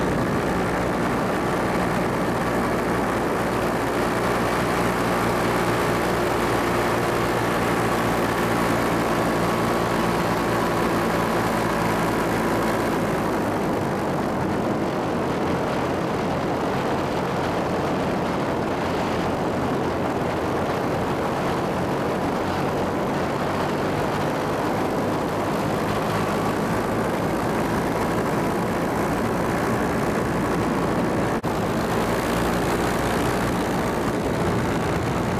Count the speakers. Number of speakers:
0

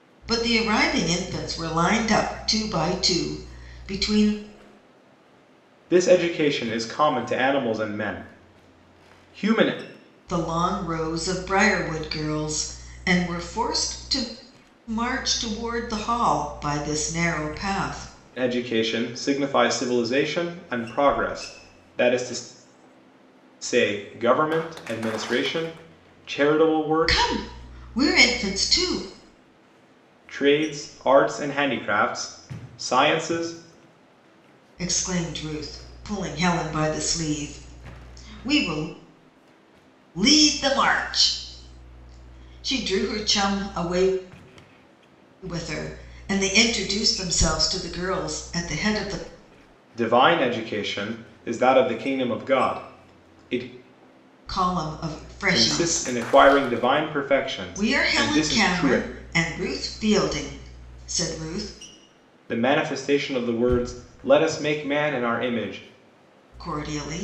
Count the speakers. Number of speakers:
2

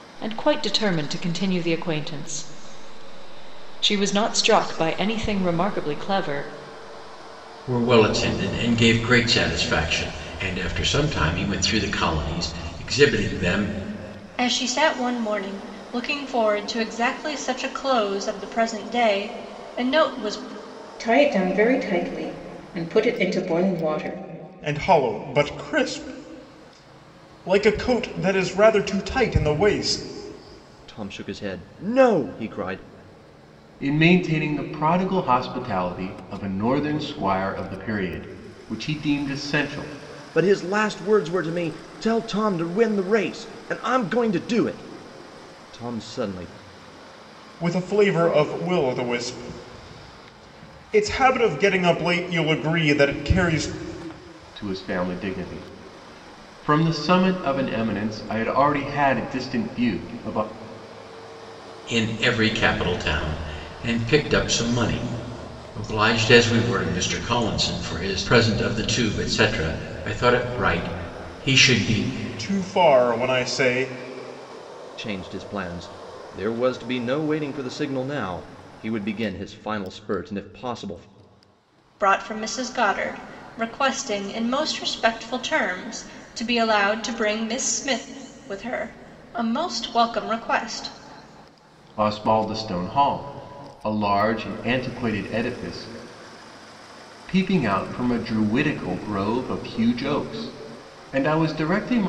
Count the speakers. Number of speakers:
7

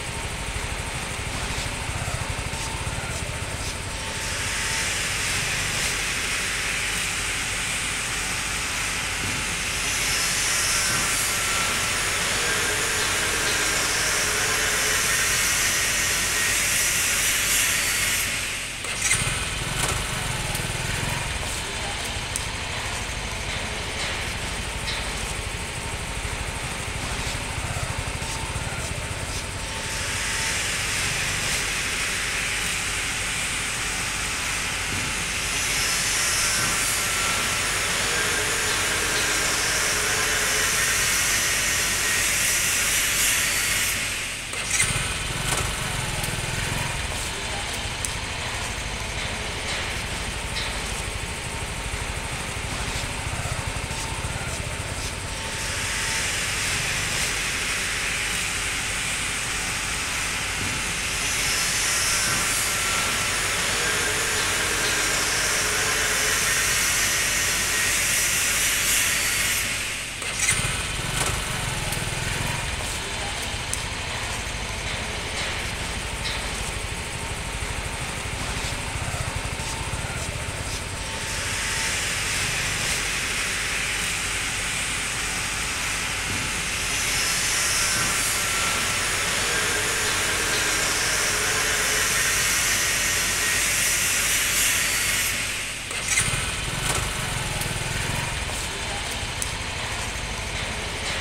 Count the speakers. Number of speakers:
0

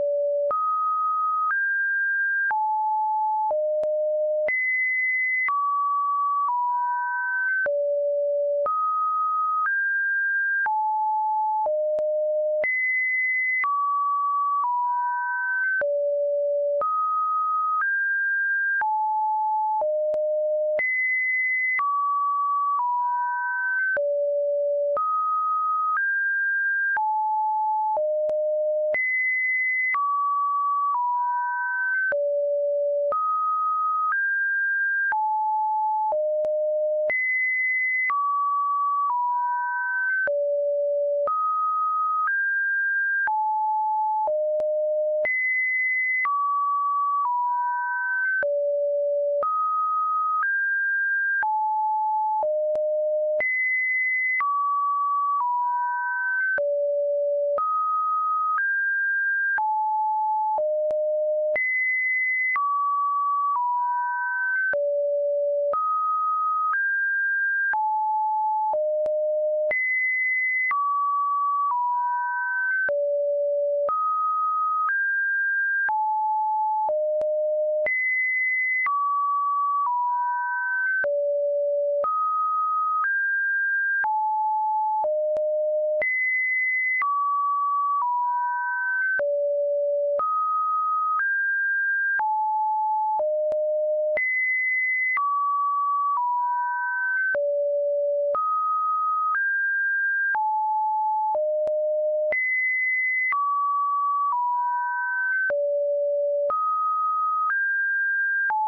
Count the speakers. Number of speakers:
0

